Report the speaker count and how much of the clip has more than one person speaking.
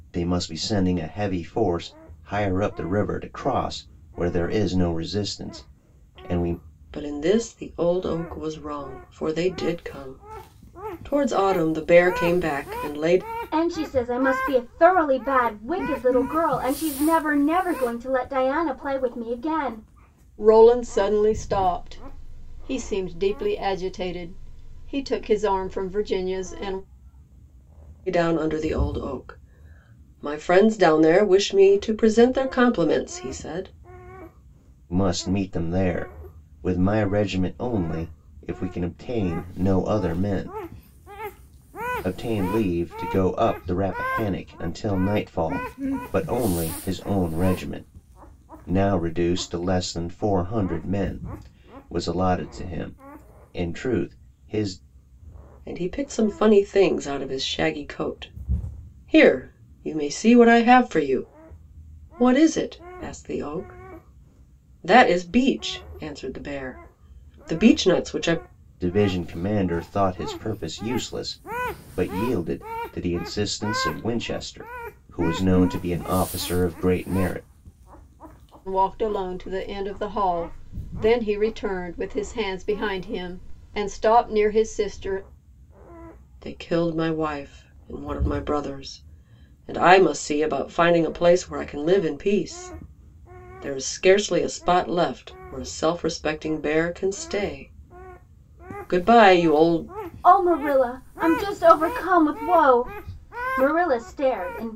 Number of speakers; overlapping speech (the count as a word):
four, no overlap